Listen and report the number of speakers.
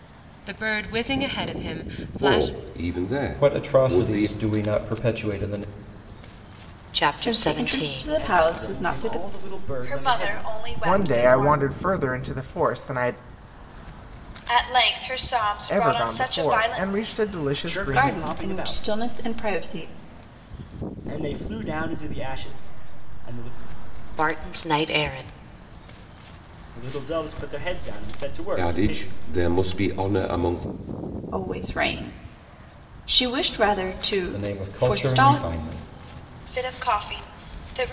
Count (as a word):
eight